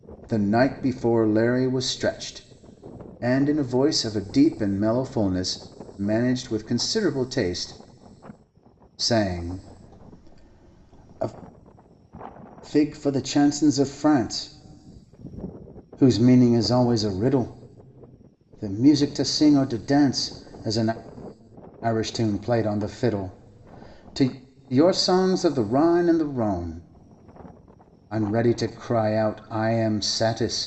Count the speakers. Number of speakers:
1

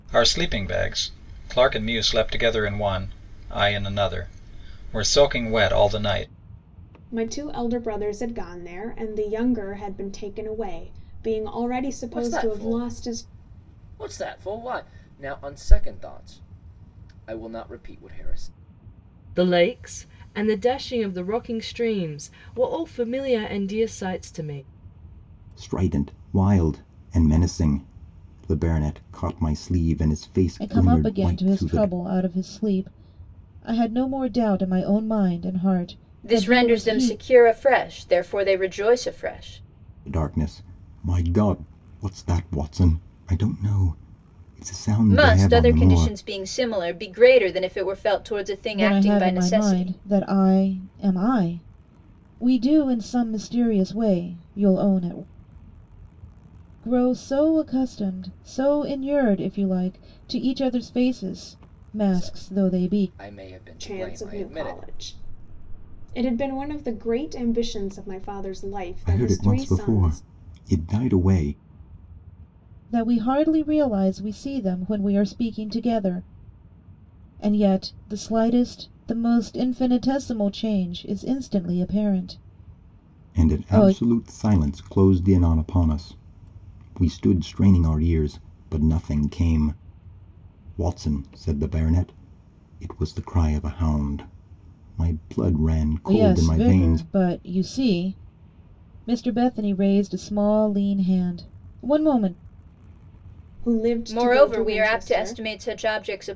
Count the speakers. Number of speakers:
7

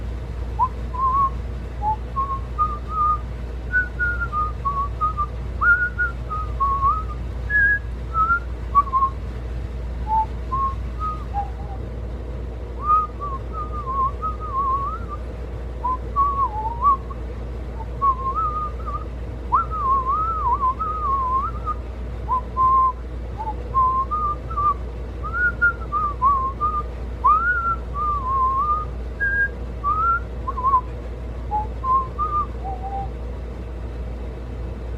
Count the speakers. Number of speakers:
0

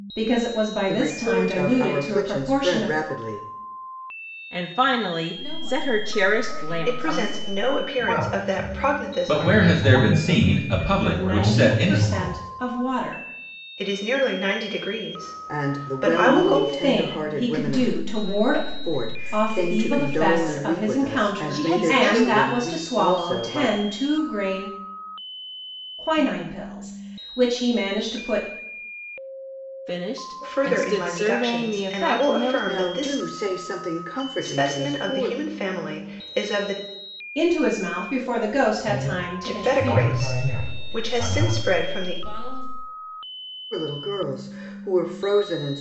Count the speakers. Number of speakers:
7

